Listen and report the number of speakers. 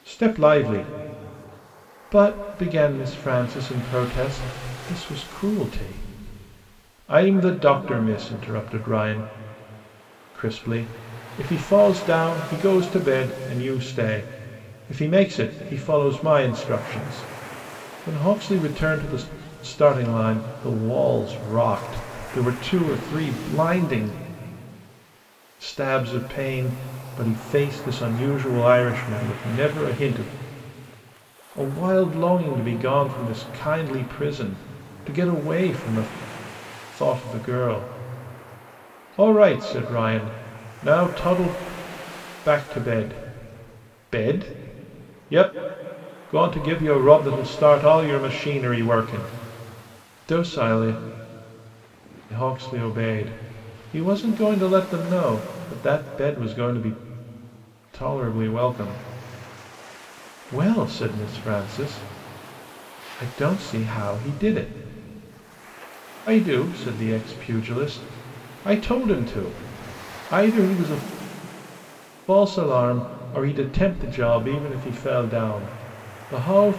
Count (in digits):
1